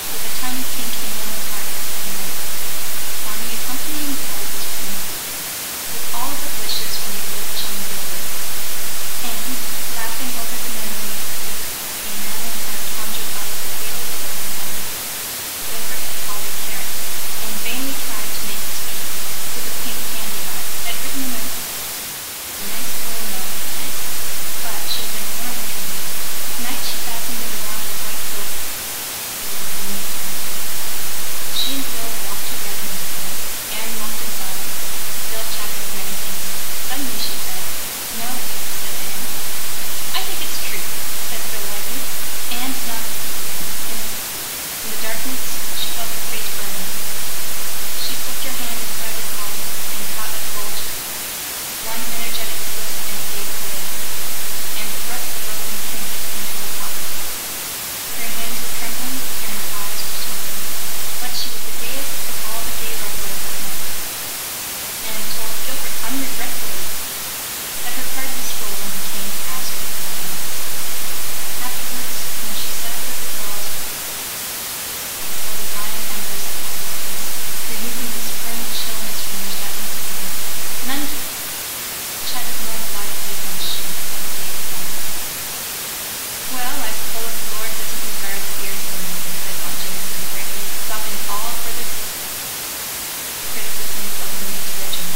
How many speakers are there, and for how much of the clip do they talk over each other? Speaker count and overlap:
one, no overlap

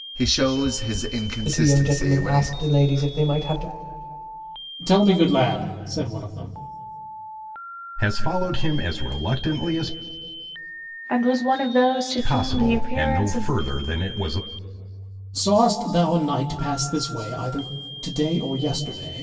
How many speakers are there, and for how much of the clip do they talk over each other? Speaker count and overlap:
five, about 13%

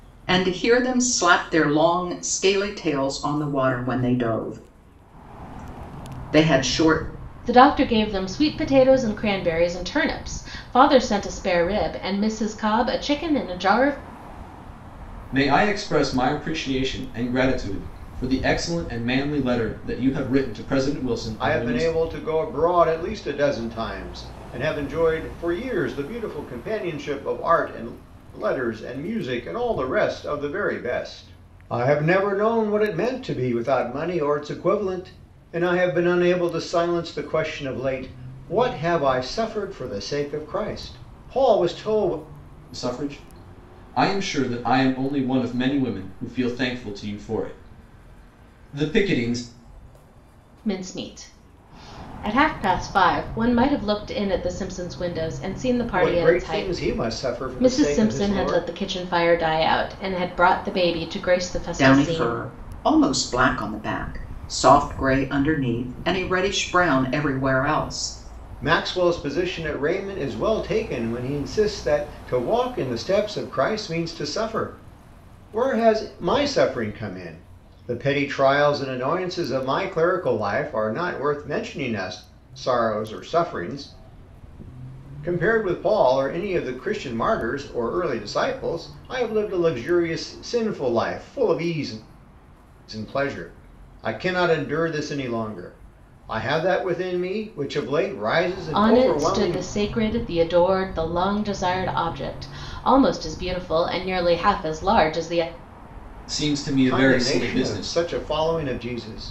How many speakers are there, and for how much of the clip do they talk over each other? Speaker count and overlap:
four, about 5%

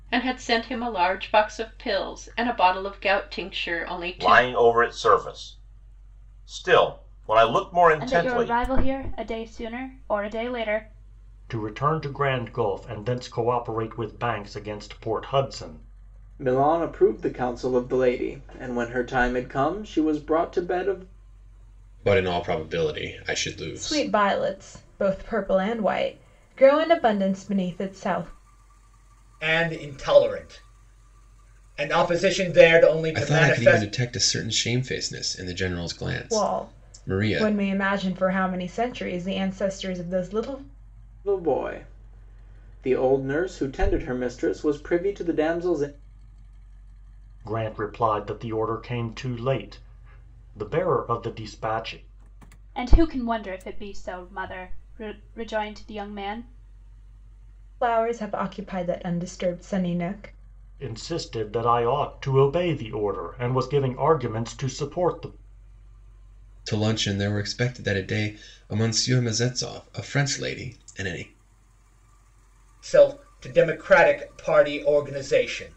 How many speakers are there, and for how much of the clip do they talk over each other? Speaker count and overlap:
eight, about 4%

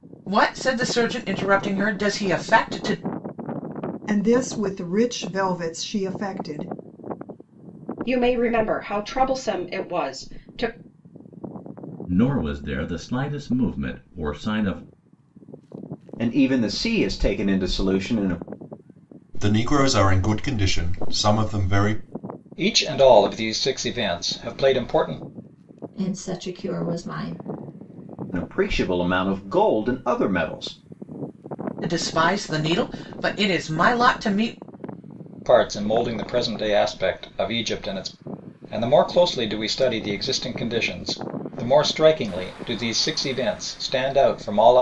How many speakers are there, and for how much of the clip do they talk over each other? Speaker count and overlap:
eight, no overlap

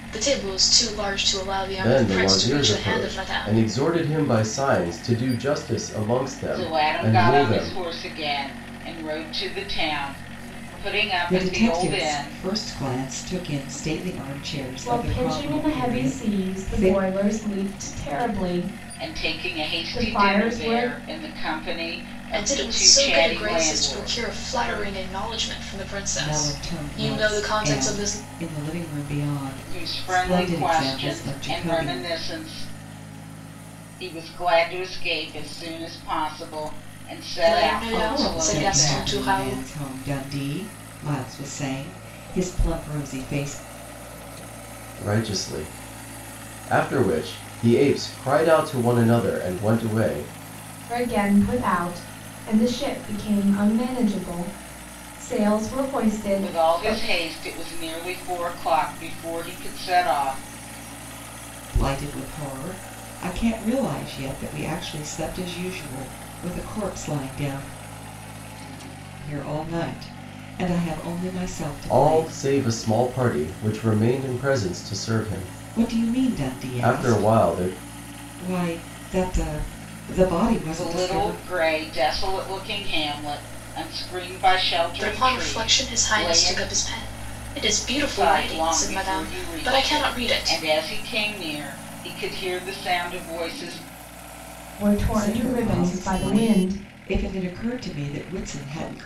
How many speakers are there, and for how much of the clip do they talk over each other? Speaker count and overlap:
five, about 28%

